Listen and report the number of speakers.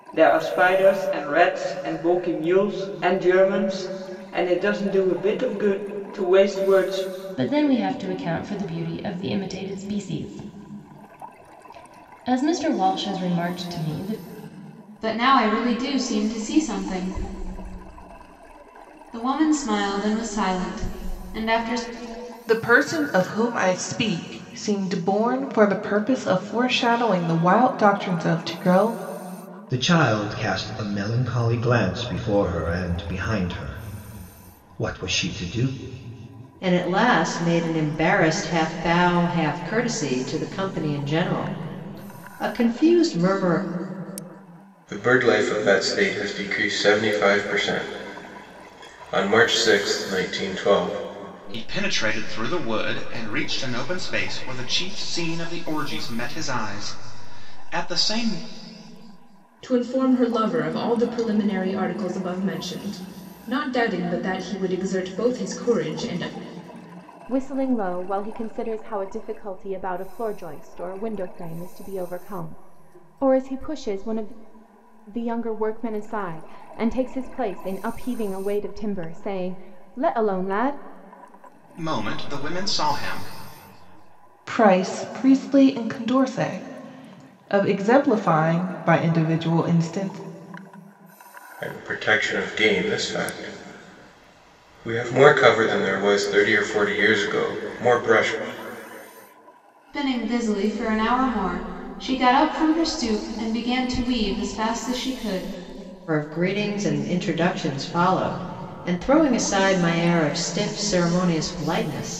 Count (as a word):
ten